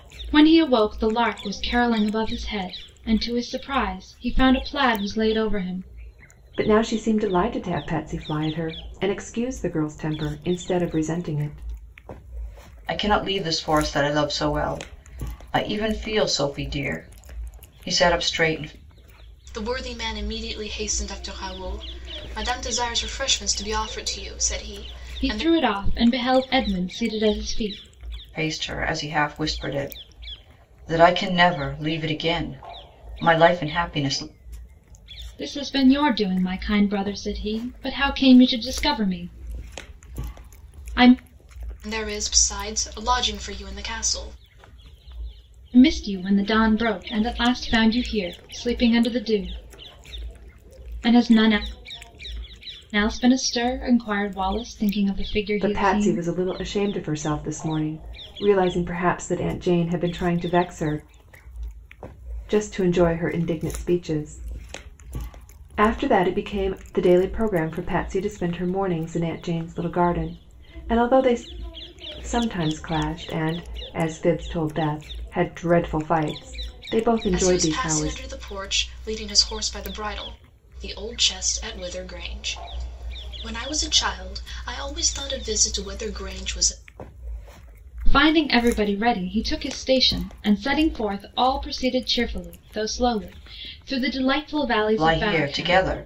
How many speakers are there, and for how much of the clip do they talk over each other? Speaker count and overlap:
4, about 3%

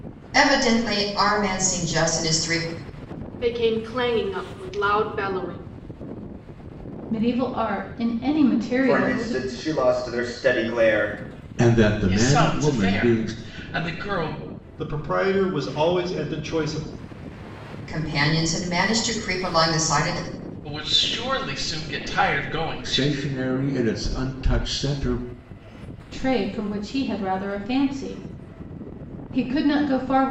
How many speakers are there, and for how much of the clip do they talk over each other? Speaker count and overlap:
7, about 8%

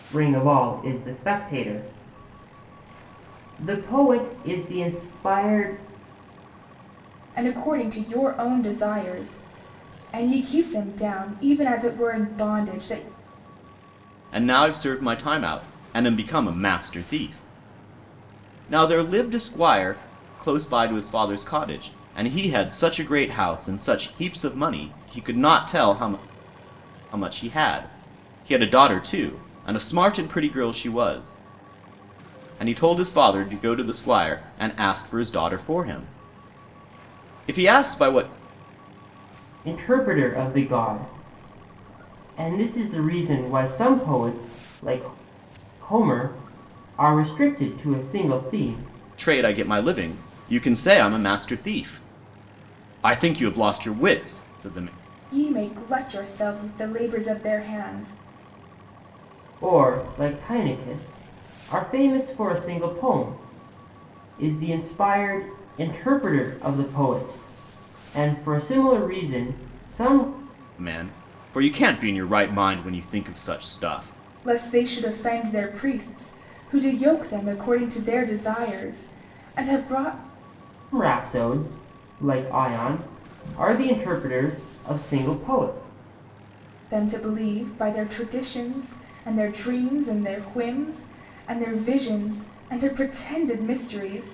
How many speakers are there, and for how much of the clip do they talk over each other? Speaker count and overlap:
3, no overlap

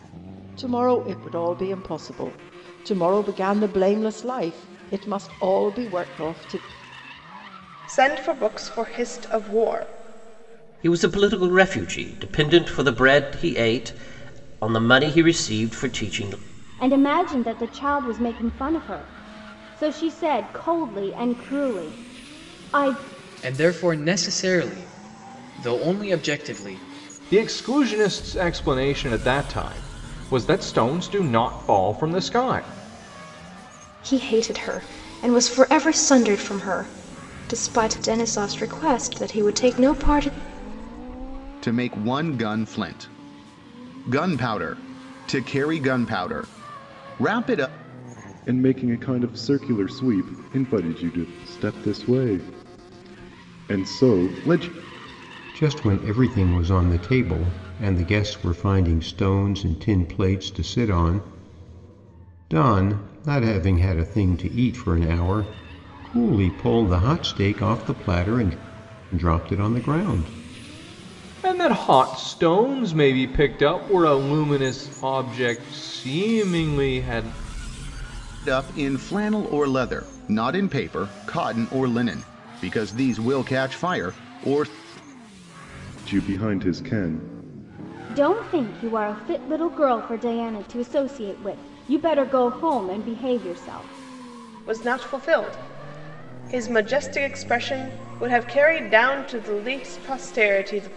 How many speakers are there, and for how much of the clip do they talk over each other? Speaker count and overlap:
10, no overlap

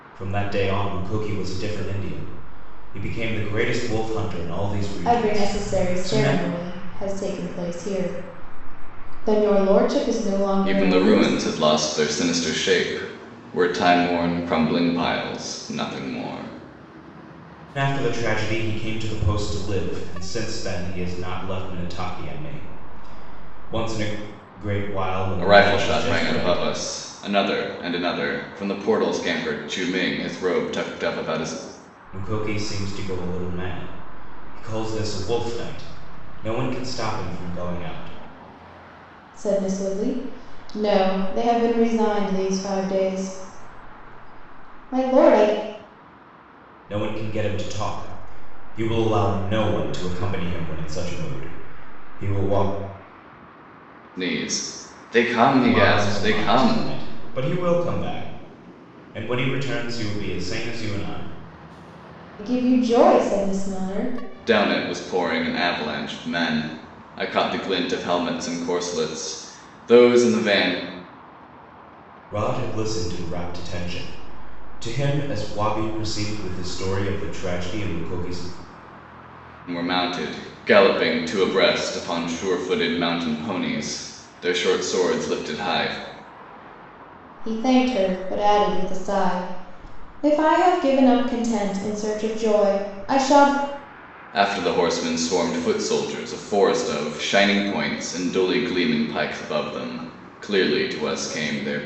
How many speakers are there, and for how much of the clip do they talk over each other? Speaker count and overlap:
3, about 5%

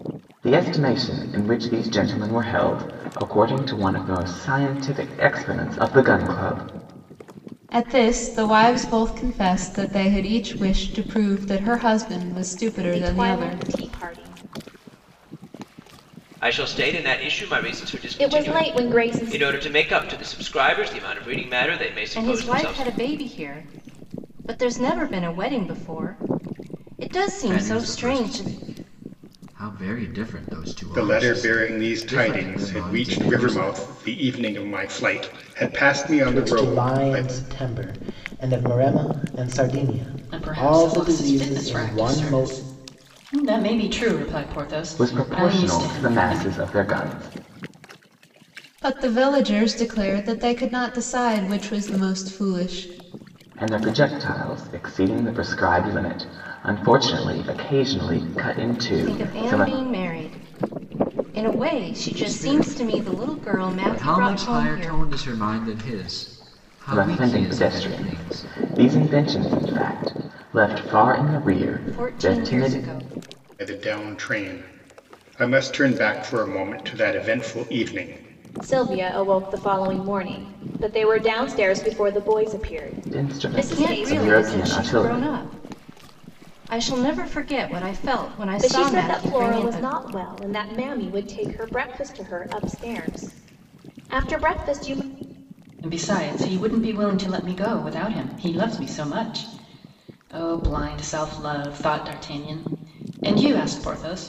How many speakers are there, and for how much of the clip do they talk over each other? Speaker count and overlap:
9, about 22%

